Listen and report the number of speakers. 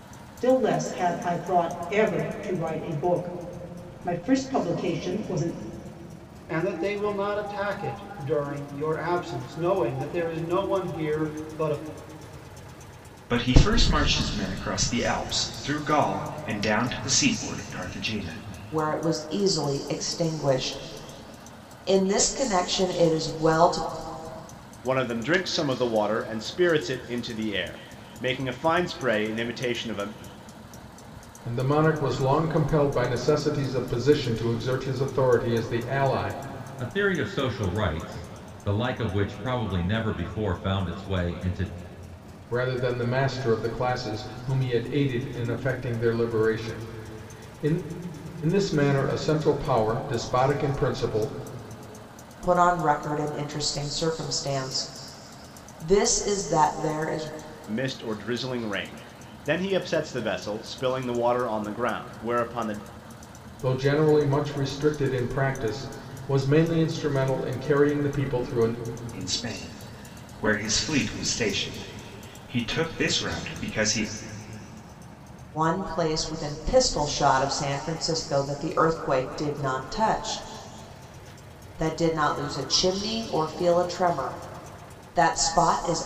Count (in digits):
7